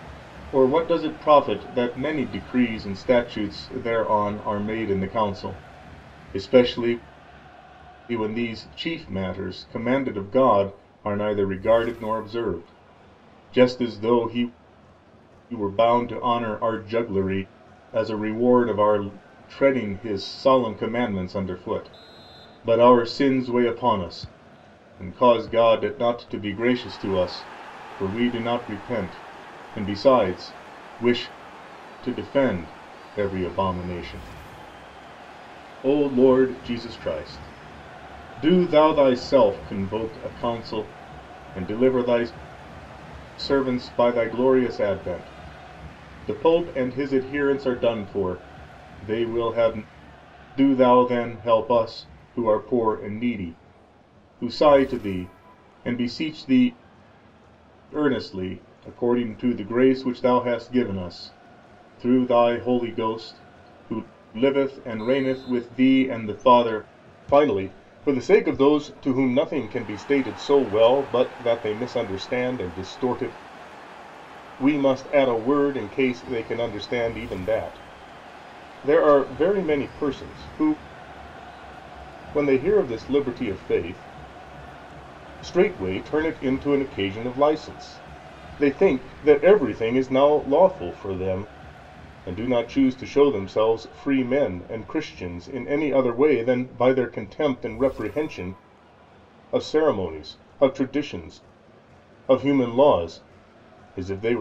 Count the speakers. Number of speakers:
one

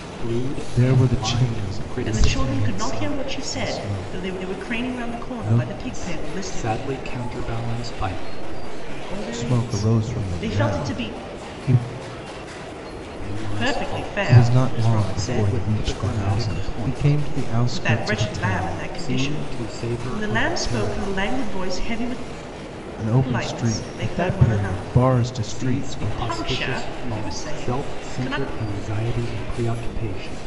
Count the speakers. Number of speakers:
three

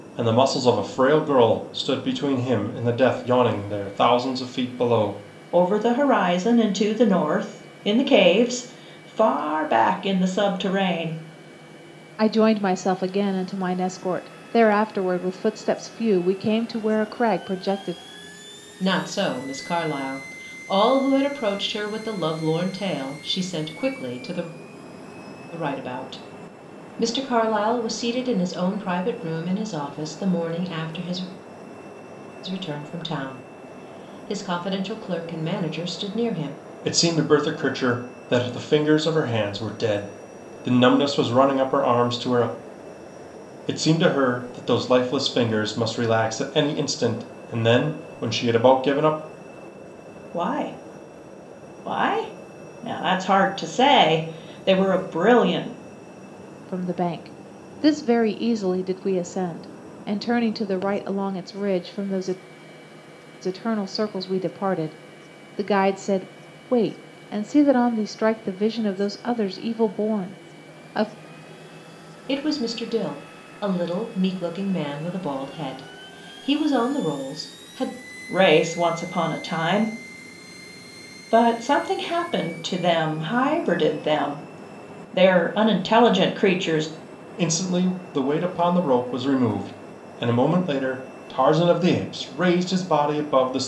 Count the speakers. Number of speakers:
four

